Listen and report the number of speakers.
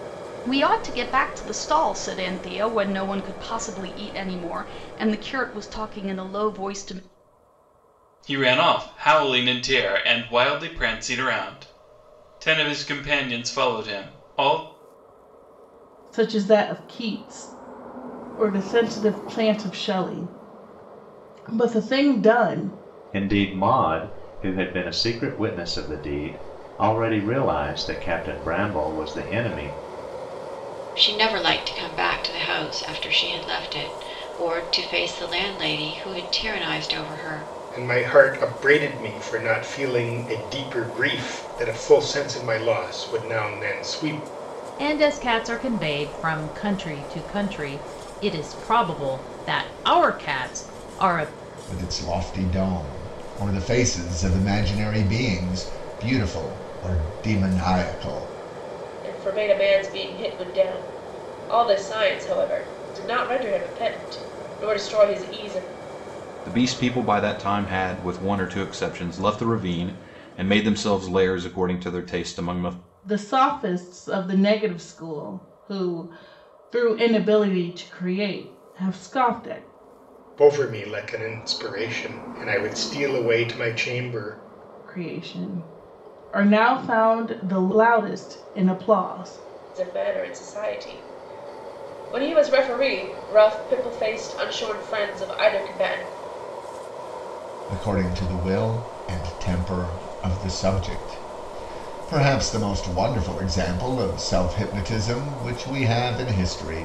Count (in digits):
10